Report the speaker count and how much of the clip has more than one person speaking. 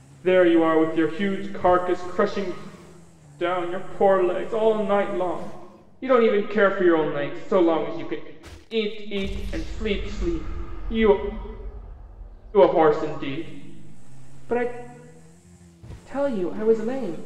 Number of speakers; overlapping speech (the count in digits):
1, no overlap